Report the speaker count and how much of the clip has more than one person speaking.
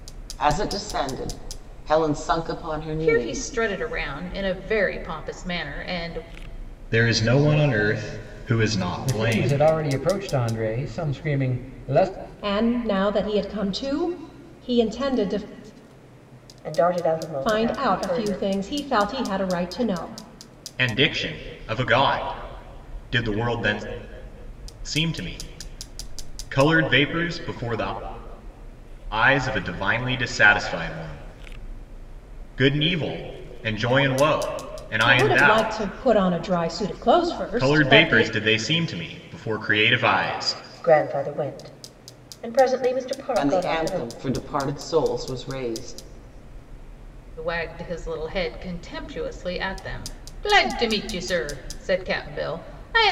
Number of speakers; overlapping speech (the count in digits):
6, about 9%